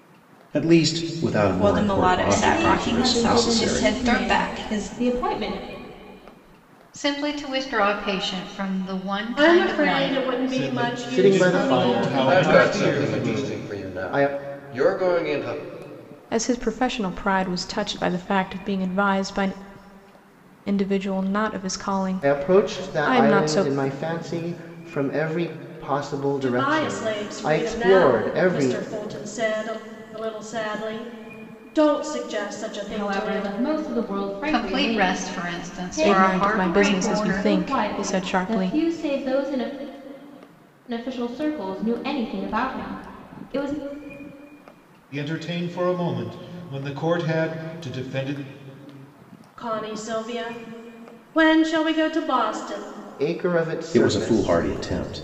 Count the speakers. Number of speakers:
9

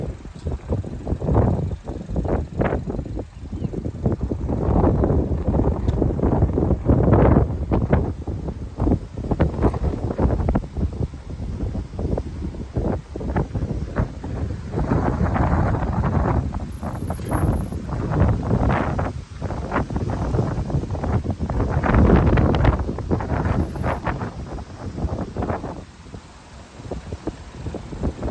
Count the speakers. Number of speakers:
0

